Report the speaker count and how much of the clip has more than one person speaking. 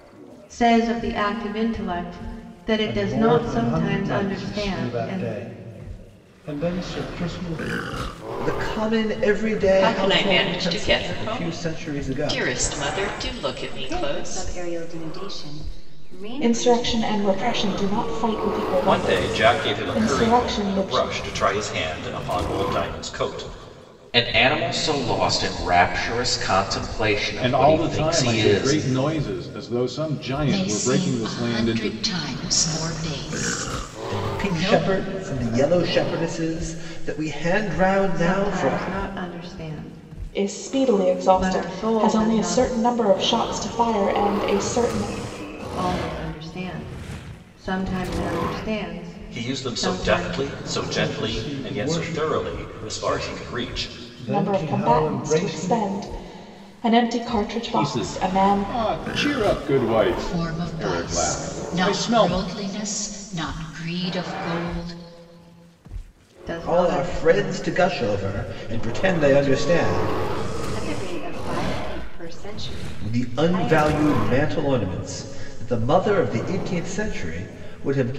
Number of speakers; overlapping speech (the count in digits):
10, about 37%